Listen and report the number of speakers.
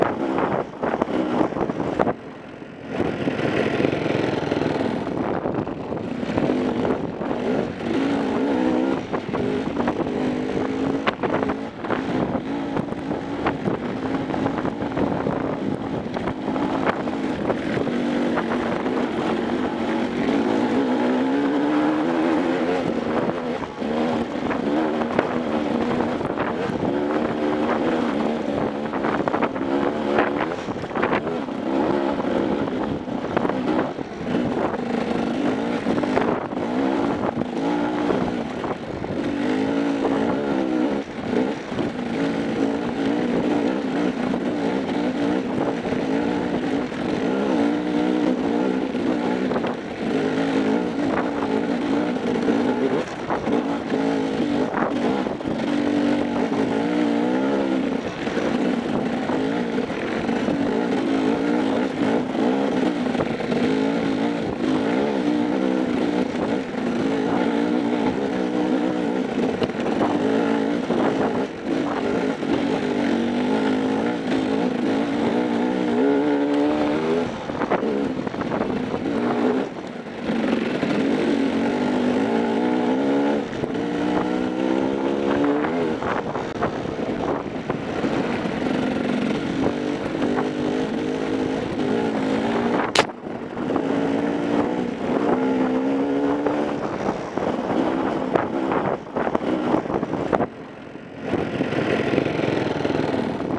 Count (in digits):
0